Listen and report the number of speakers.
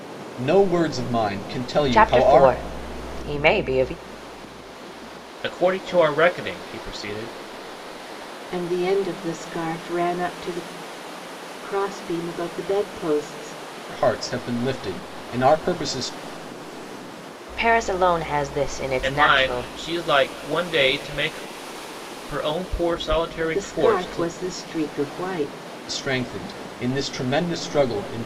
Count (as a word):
four